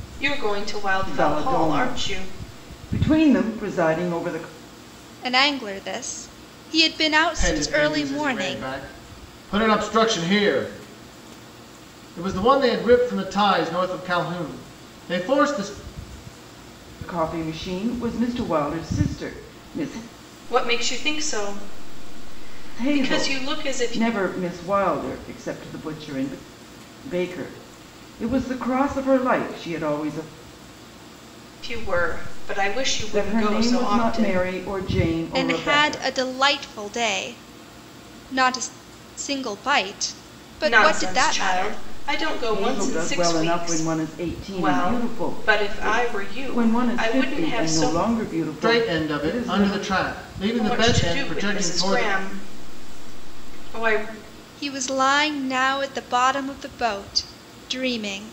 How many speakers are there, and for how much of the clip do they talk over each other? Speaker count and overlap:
four, about 25%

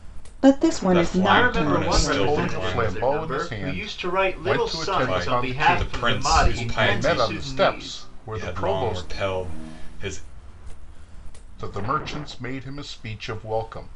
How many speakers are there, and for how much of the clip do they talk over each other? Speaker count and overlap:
four, about 54%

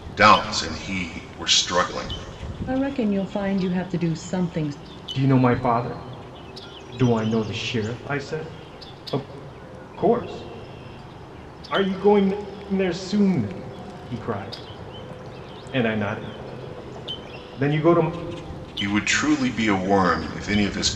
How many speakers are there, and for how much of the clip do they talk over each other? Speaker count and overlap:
three, no overlap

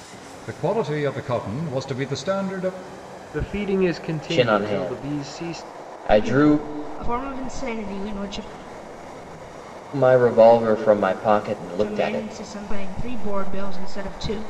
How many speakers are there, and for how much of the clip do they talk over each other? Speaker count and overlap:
four, about 18%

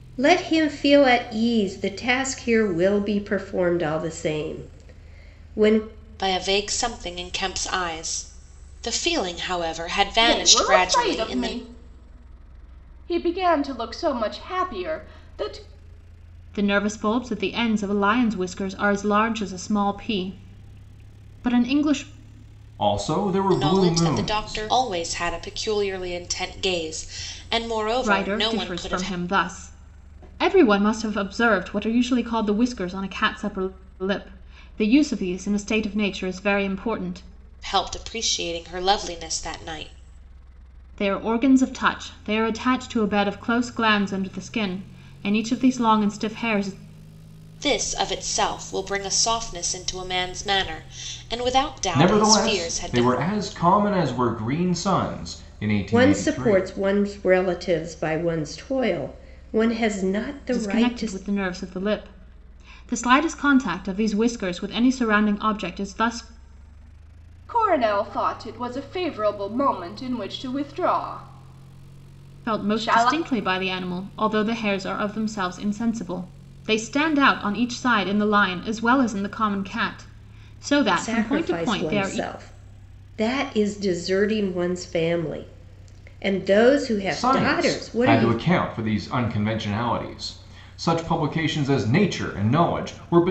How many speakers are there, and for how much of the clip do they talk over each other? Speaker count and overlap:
five, about 10%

